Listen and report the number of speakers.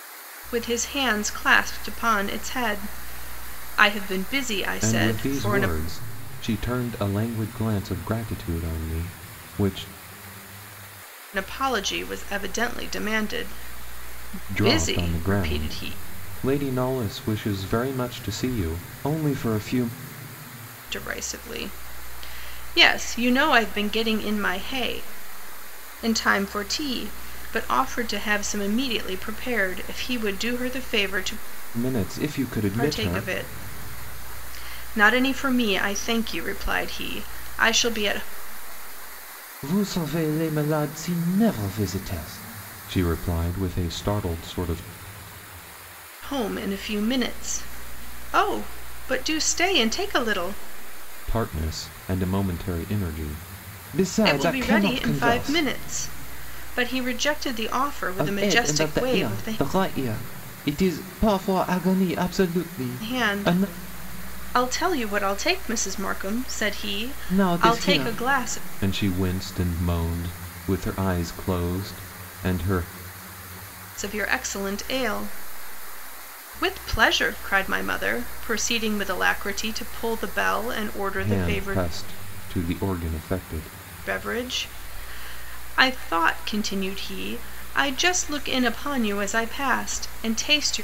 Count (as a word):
two